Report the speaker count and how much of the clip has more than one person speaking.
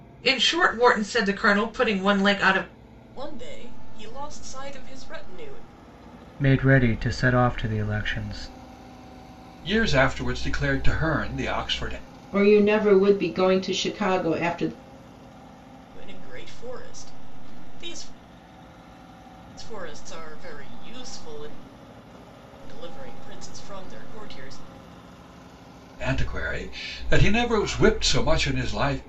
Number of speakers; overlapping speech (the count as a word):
five, no overlap